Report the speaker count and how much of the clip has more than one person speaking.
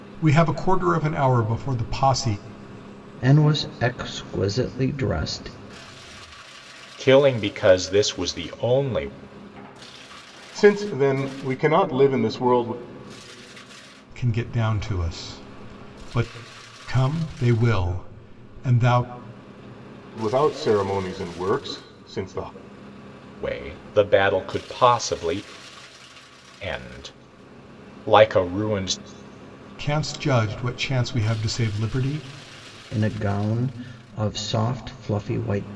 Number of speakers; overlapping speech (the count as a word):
four, no overlap